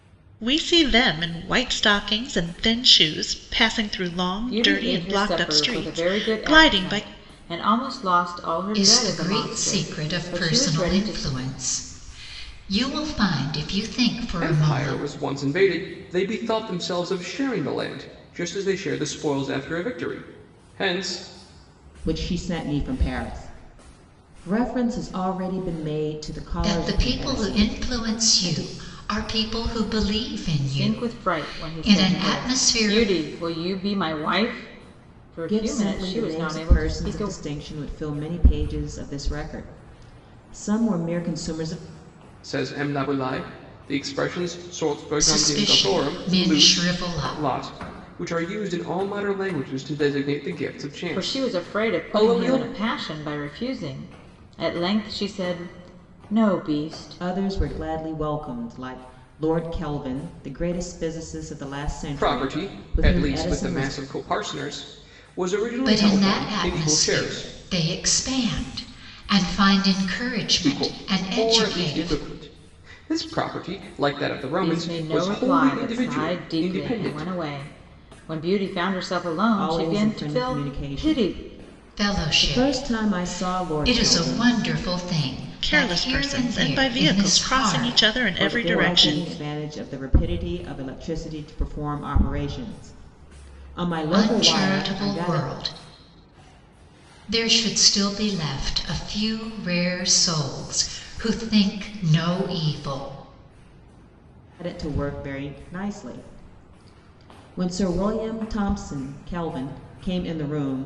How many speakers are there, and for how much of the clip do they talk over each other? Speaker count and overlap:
five, about 31%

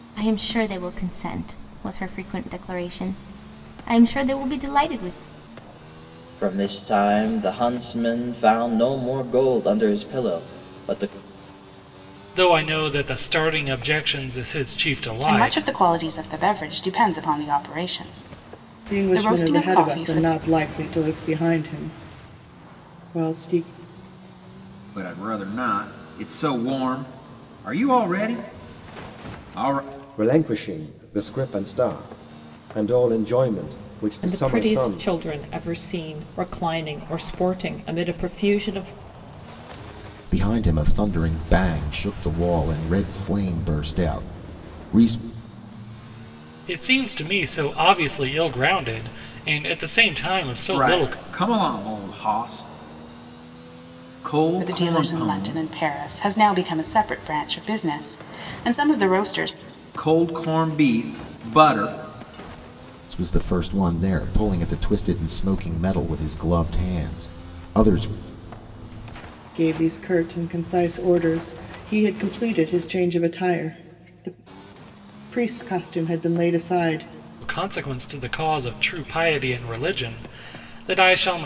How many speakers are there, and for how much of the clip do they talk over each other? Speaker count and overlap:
nine, about 5%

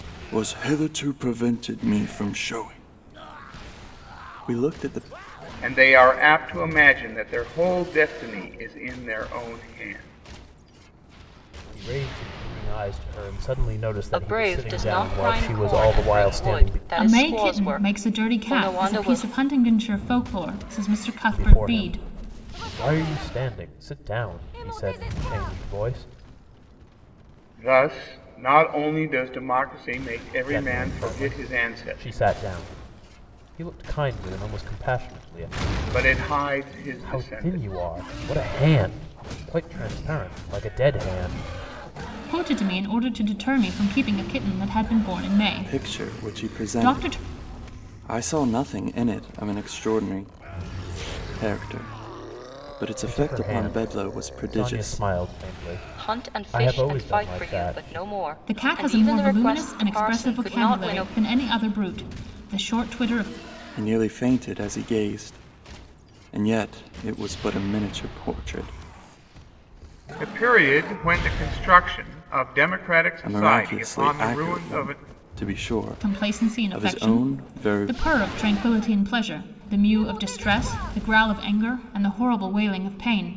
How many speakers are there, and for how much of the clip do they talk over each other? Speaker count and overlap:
five, about 25%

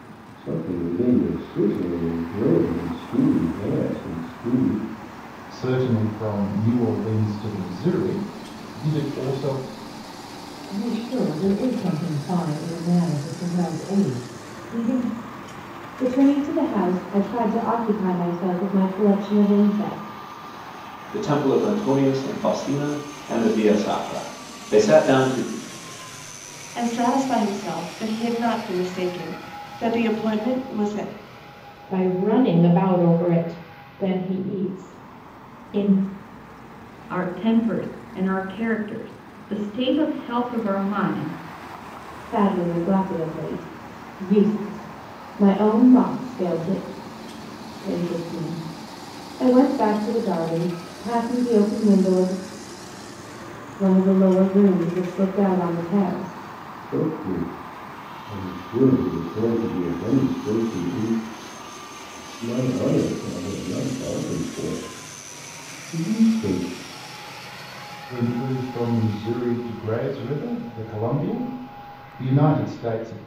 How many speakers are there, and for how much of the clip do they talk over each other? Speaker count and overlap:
eight, no overlap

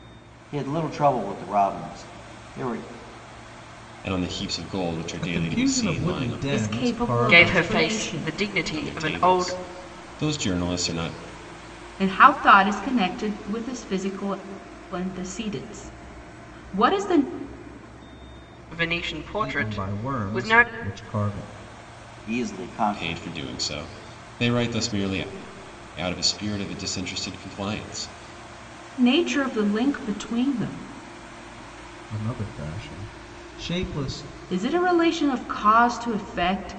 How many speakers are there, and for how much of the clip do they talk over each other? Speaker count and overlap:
five, about 15%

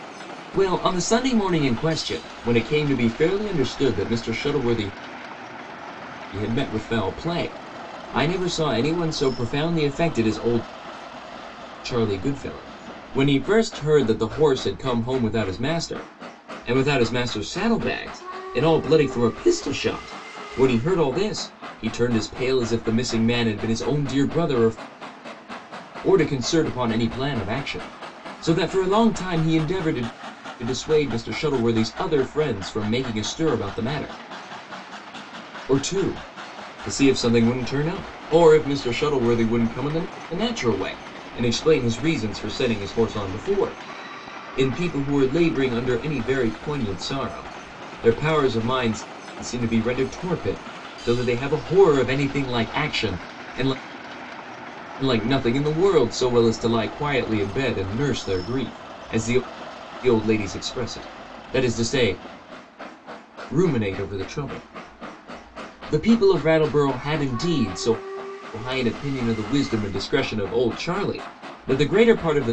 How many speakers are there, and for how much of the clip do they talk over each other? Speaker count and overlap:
one, no overlap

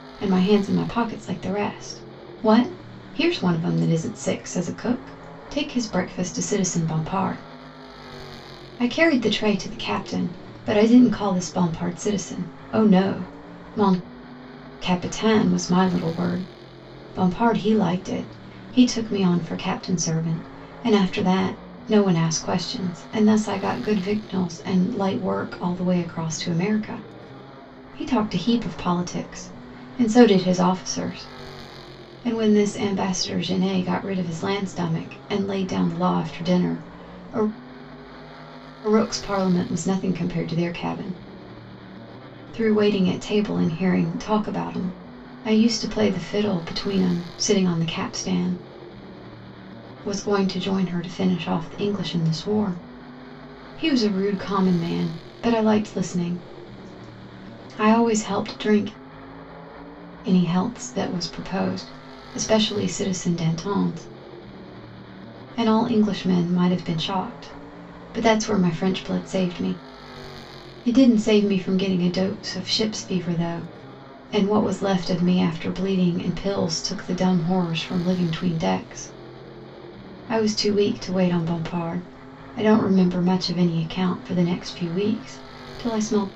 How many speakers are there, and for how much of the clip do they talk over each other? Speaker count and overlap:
one, no overlap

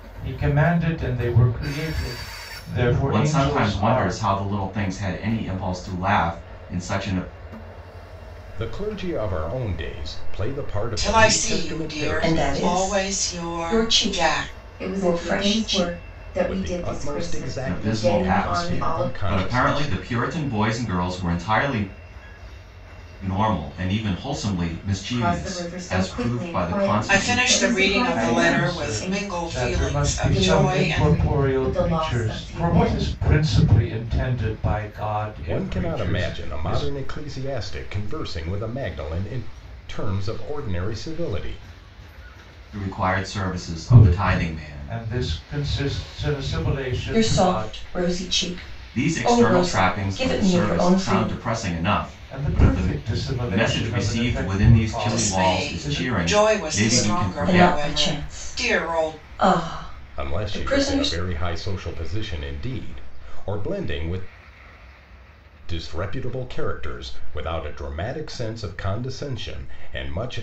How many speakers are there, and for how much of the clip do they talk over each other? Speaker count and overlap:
six, about 44%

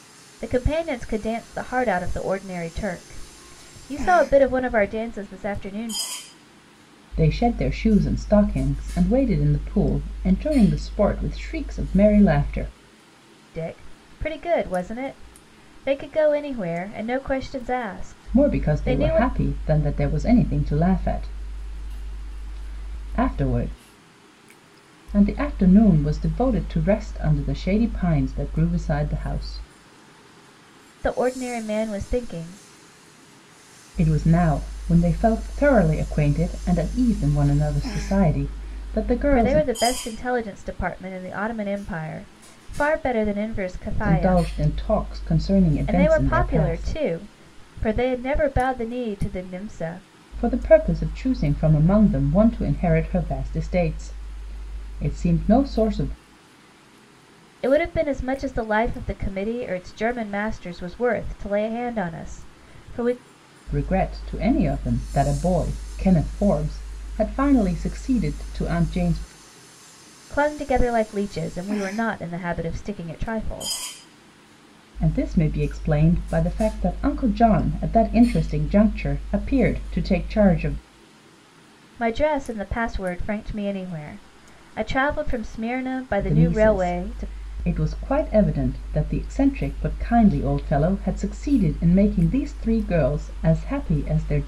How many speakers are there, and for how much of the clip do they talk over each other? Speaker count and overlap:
two, about 4%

